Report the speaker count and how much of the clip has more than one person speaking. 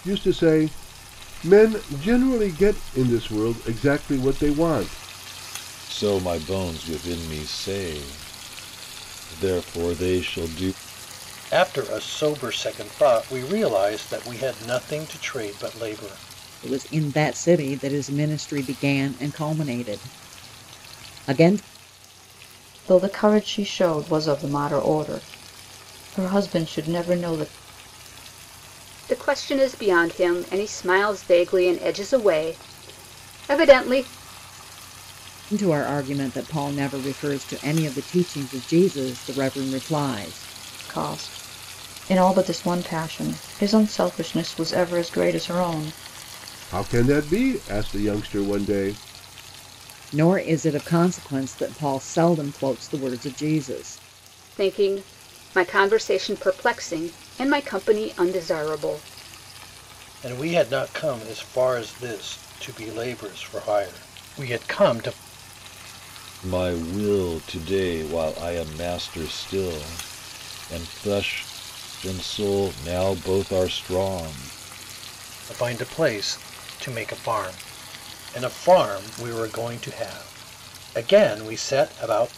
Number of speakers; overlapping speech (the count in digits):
6, no overlap